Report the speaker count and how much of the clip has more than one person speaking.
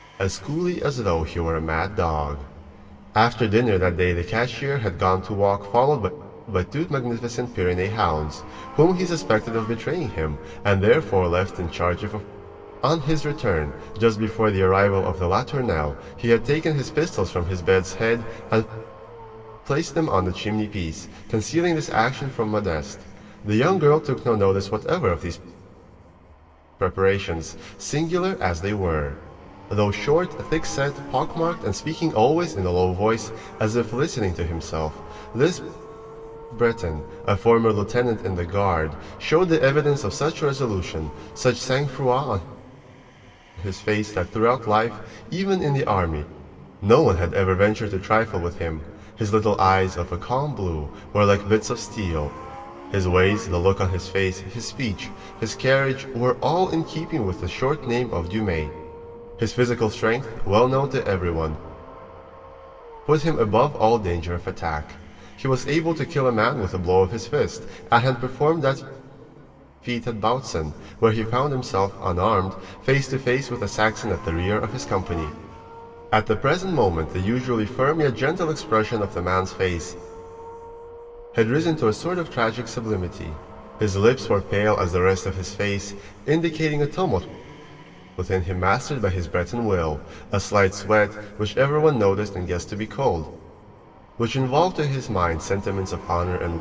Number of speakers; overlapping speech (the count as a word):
one, no overlap